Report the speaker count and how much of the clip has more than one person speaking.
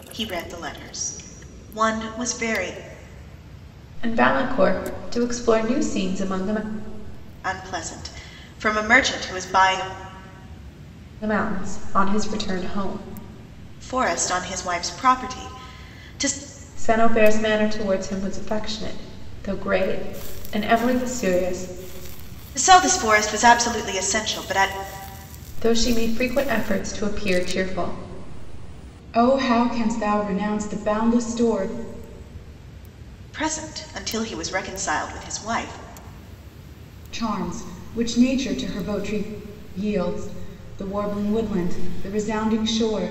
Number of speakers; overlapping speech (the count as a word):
two, no overlap